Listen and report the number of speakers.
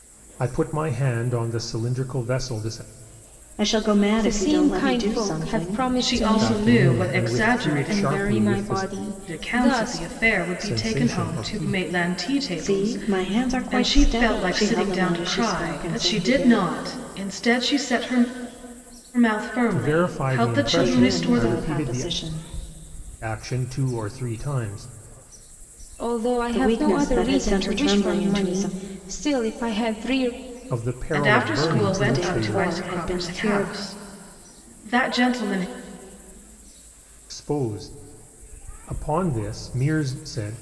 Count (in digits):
4